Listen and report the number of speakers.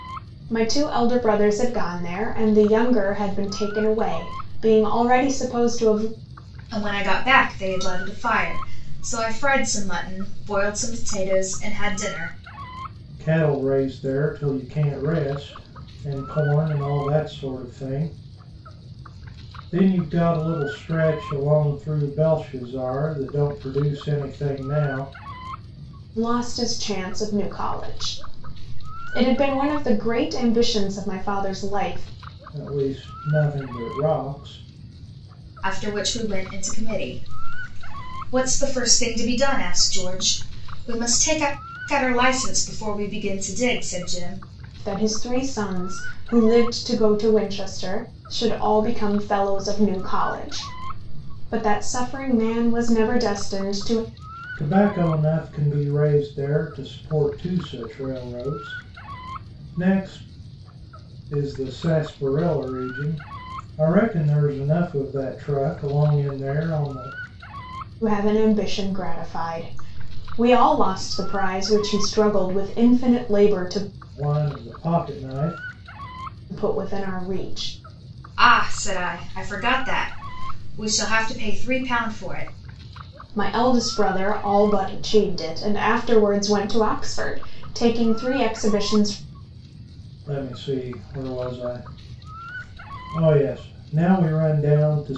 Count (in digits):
3